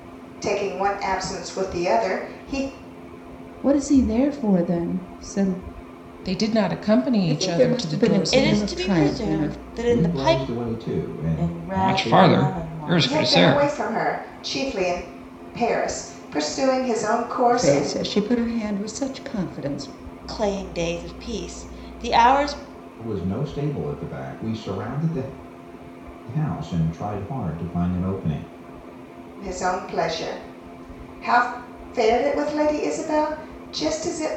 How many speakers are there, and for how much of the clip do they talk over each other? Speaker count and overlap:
8, about 17%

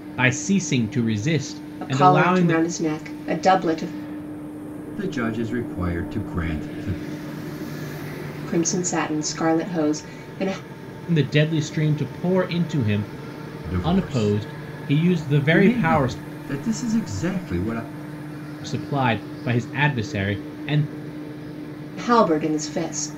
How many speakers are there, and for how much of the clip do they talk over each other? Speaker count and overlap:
3, about 9%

